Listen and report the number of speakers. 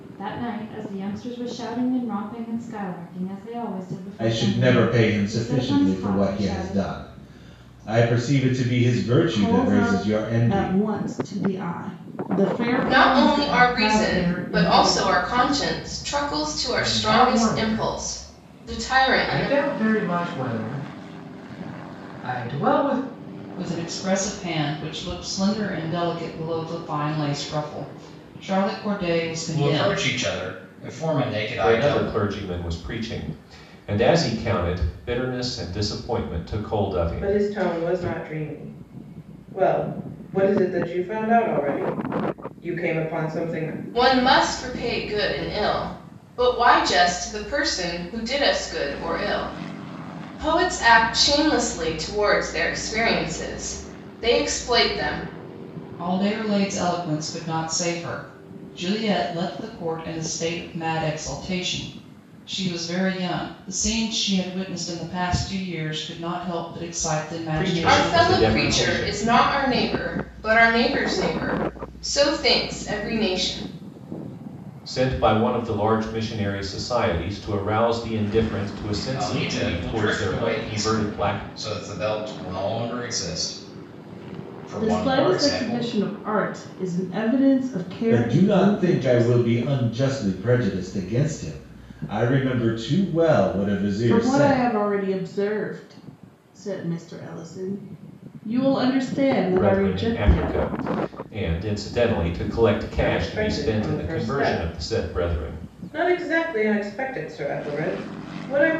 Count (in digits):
9